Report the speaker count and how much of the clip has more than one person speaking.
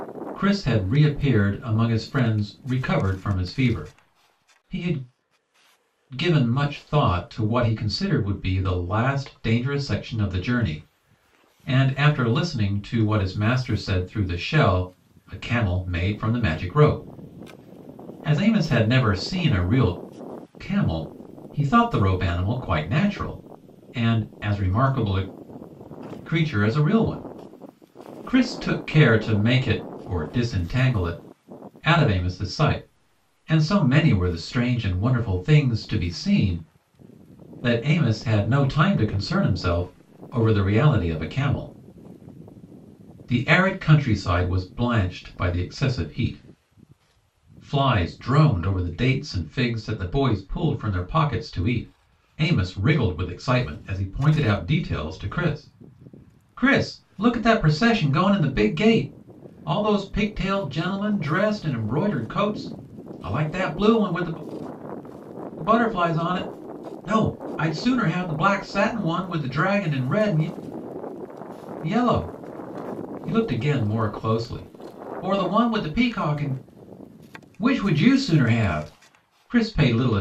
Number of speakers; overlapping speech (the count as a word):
one, no overlap